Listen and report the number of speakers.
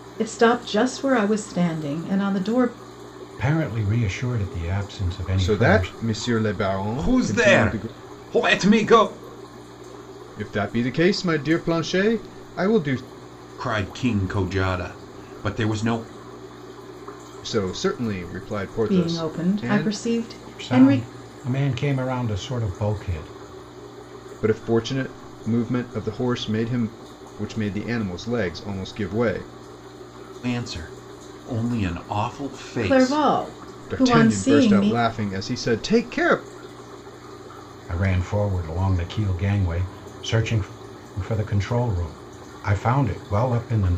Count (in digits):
4